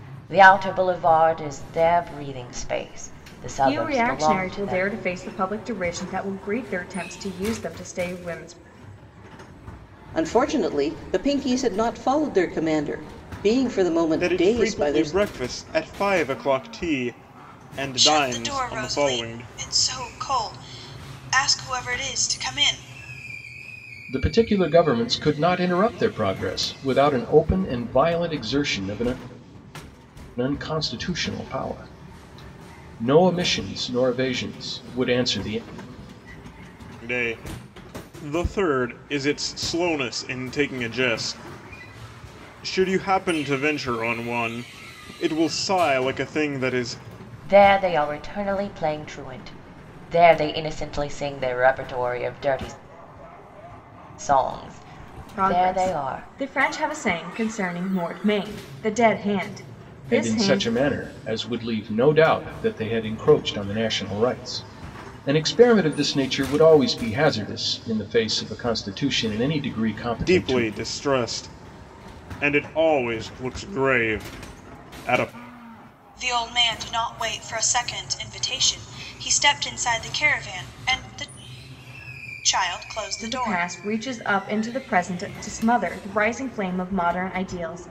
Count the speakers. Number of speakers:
6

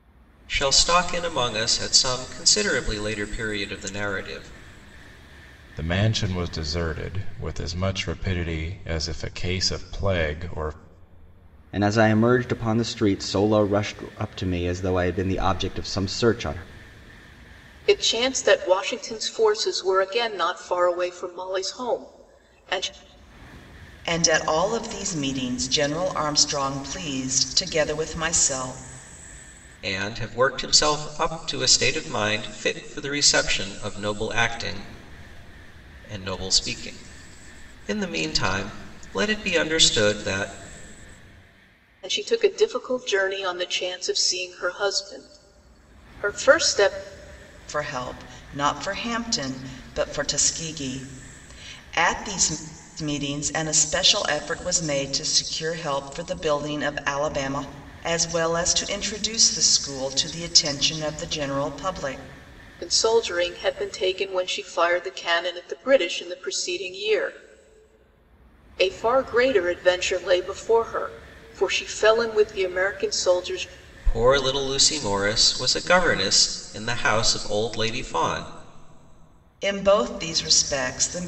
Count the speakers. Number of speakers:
5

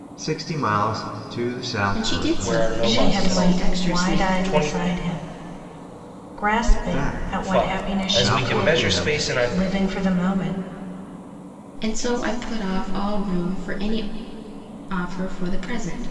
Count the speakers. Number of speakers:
4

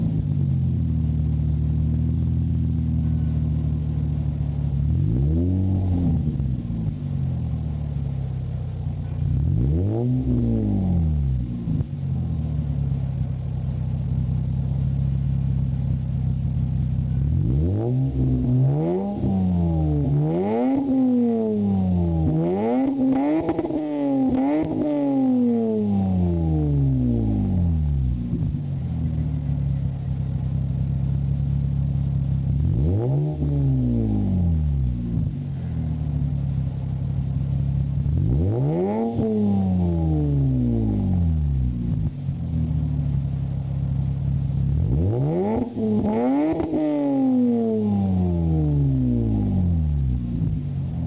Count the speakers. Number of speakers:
0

